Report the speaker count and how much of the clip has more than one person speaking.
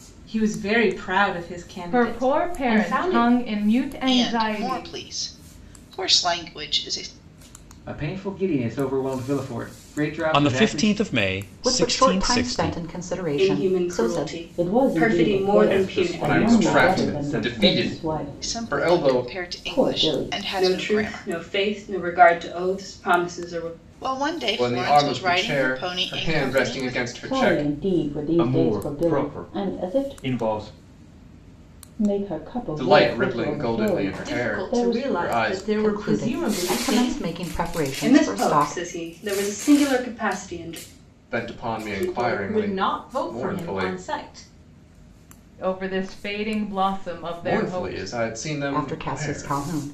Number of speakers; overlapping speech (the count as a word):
ten, about 51%